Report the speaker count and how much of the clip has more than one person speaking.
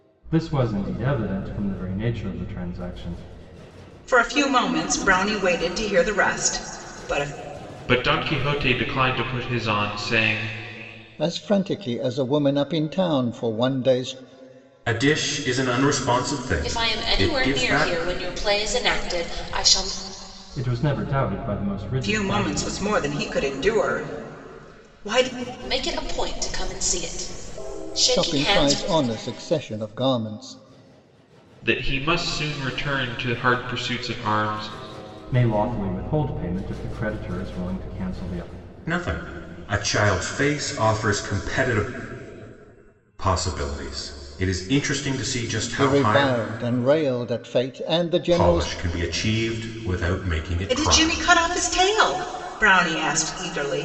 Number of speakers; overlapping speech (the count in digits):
6, about 9%